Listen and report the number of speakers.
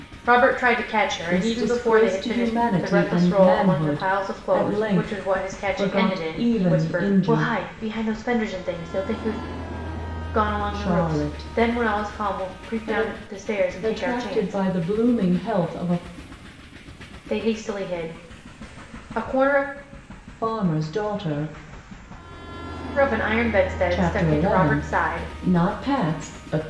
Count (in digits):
2